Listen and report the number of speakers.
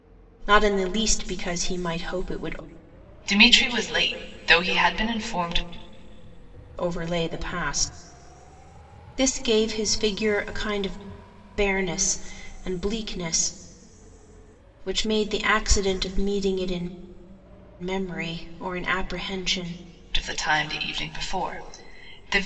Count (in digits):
2